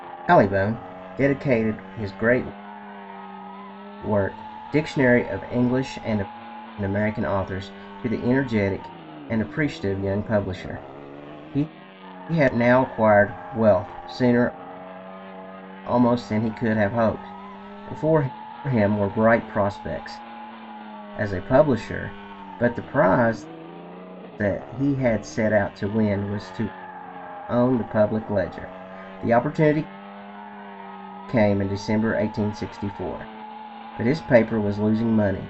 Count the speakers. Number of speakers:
1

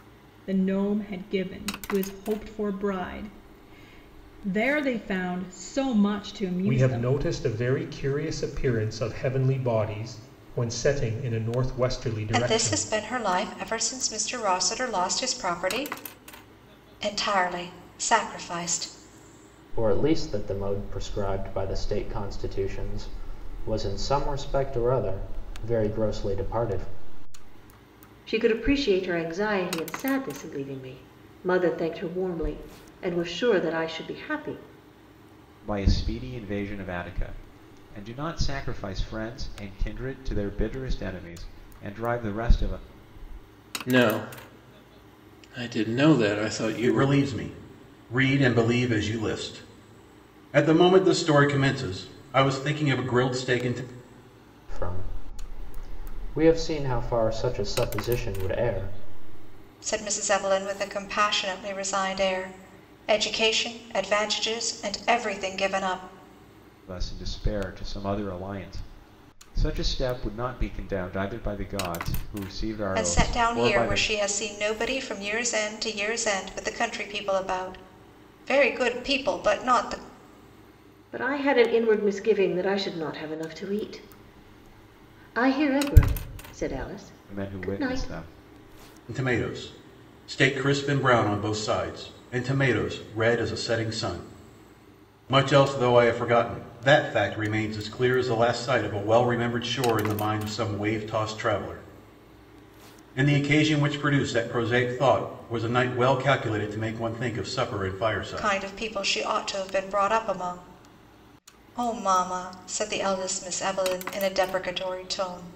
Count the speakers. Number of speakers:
8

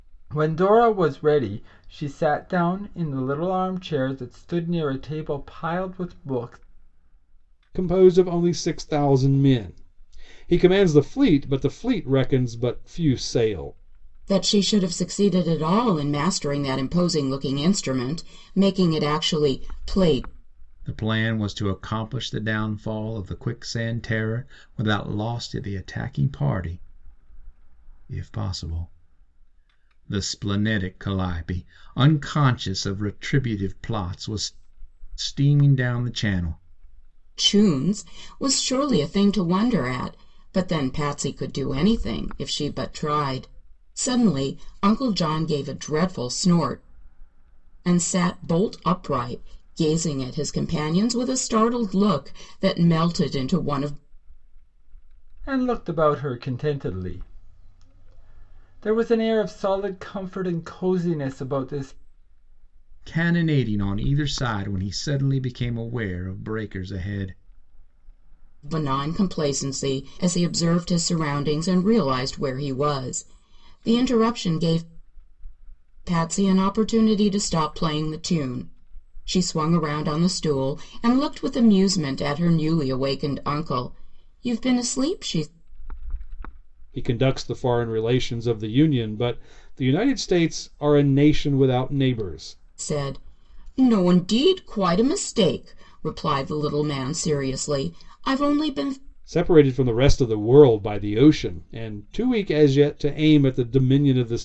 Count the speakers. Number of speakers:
4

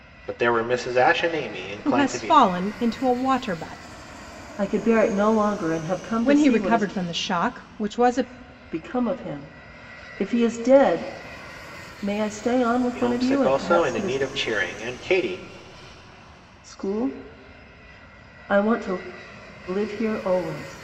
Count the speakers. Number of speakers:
3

